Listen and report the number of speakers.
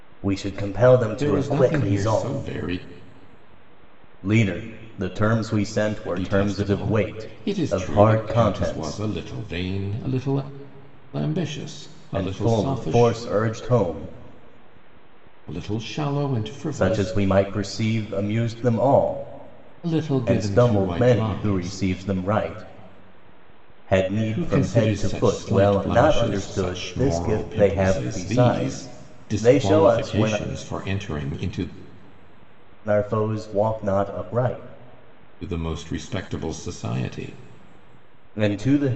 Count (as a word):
two